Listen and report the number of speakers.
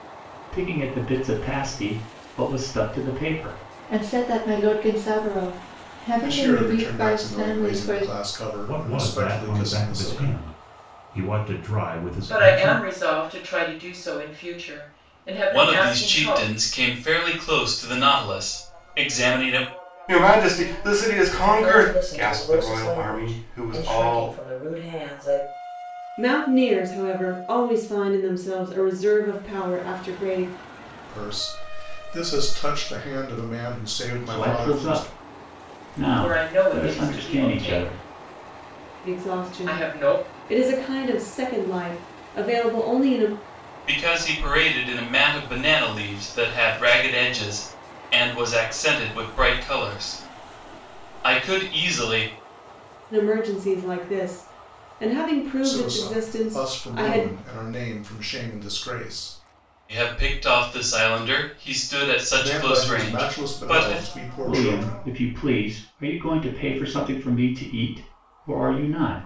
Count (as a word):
nine